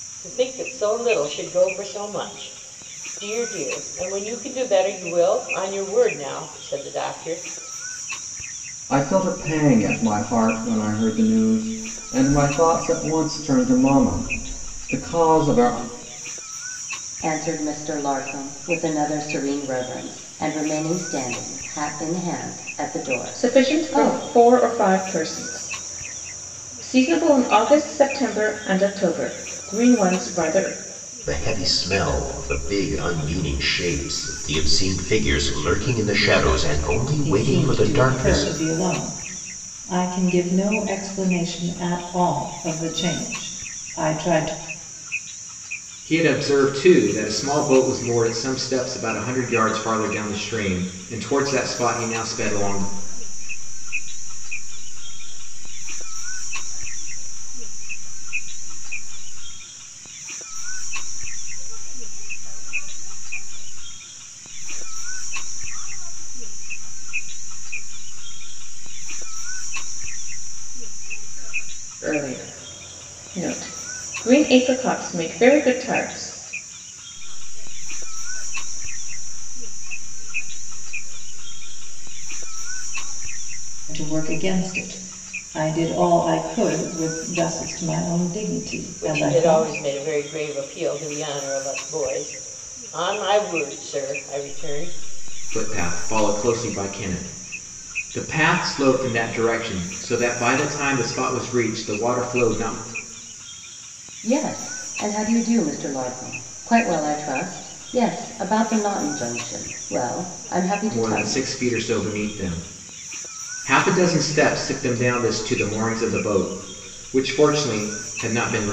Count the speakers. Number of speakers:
eight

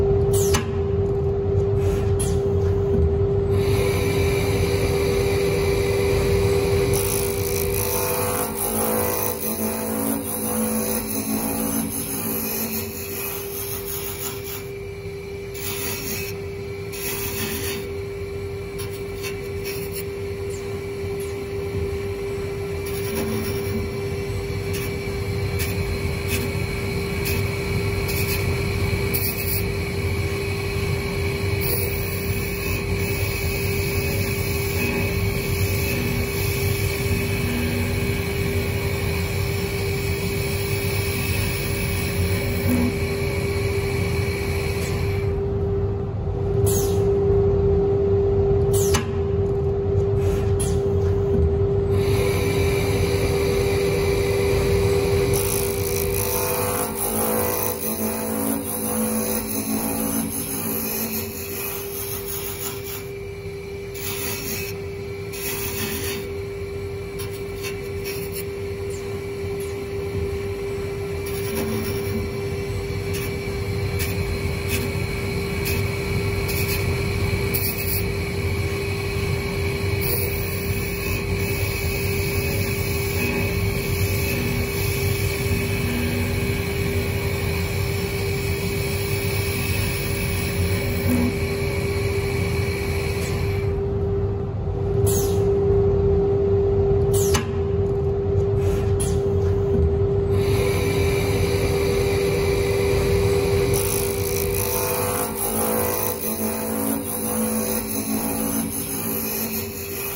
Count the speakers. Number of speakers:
zero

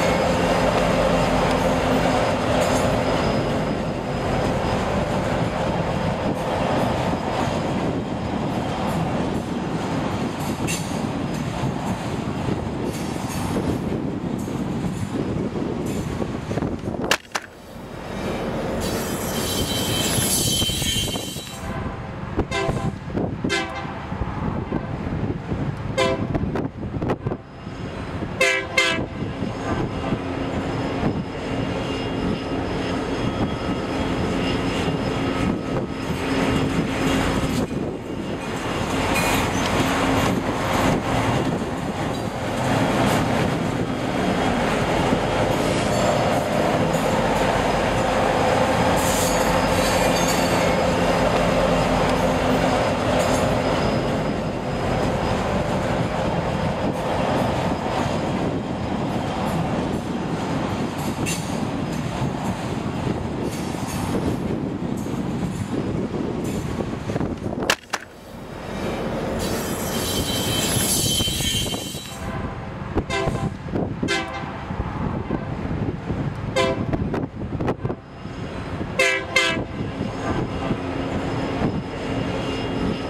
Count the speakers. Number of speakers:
zero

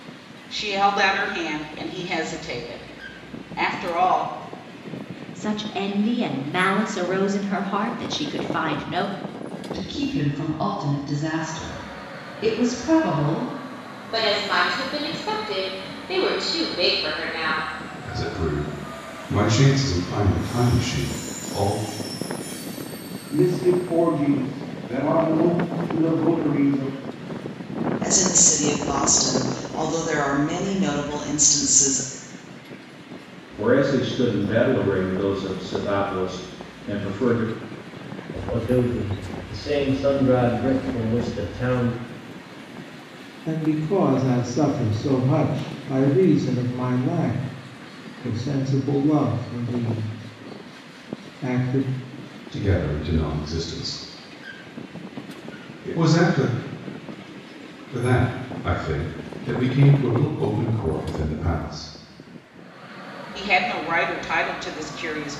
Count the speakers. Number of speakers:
ten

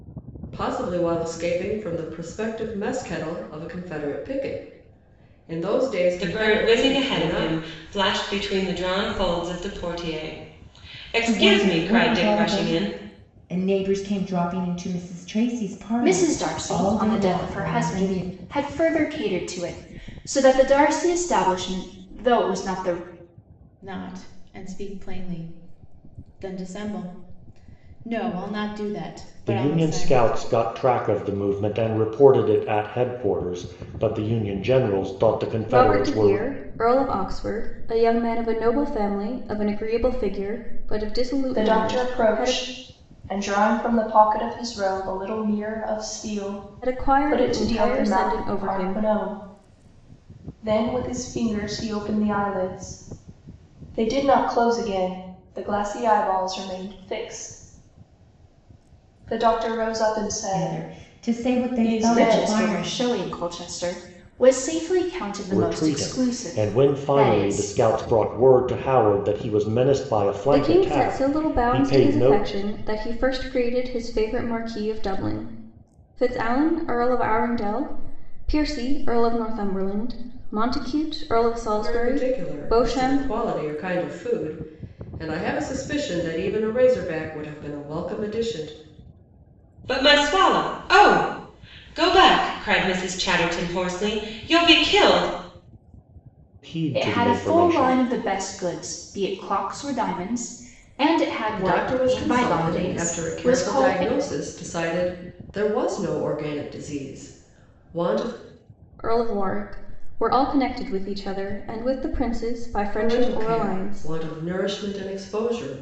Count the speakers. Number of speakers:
eight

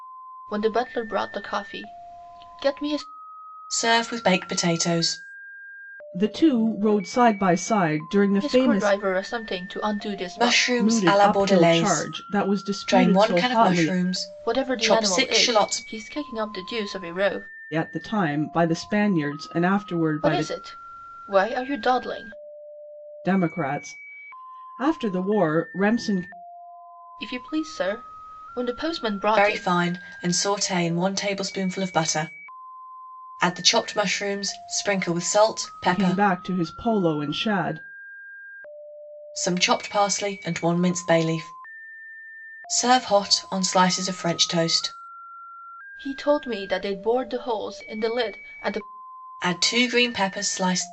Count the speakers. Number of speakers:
three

